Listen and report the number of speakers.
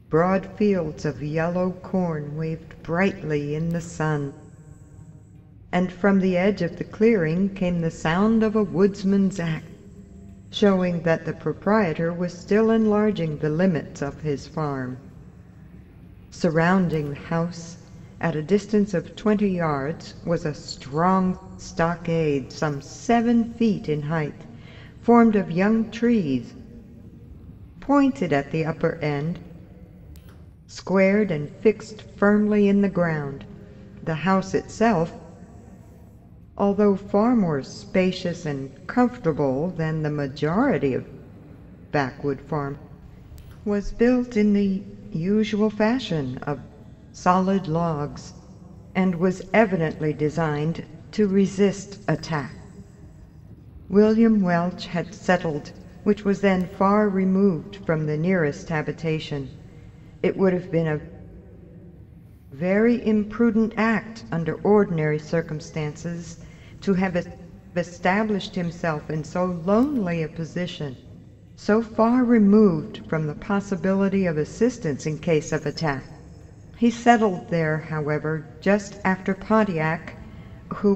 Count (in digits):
1